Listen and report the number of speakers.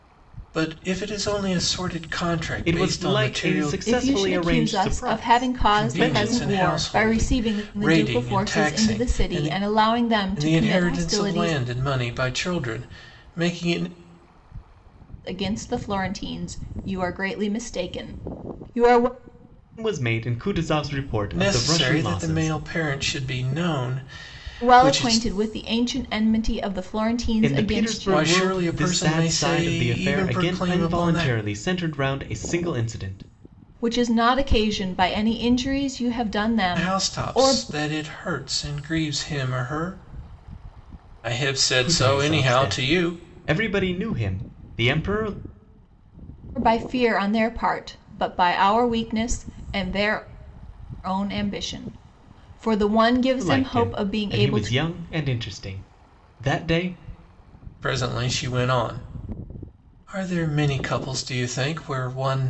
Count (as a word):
three